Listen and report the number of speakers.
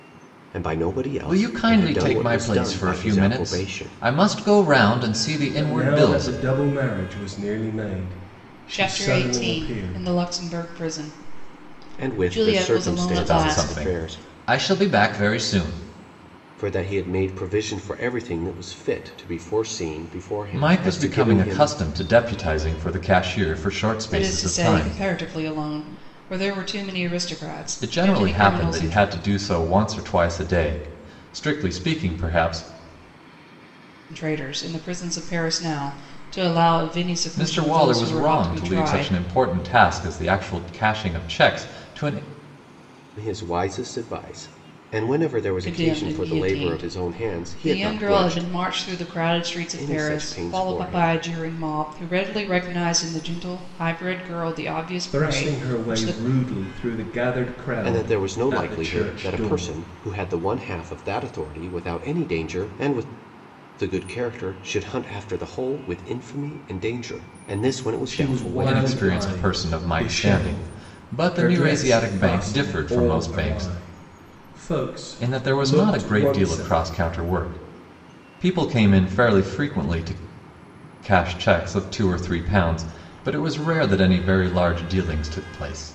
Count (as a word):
four